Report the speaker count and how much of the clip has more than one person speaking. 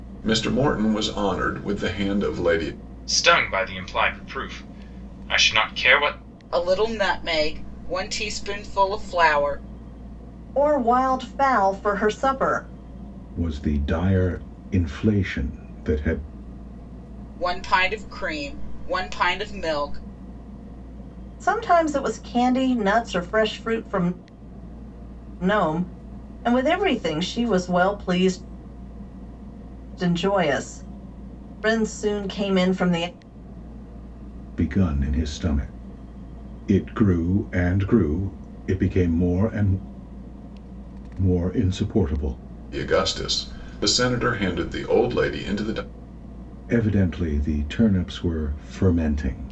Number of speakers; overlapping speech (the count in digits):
5, no overlap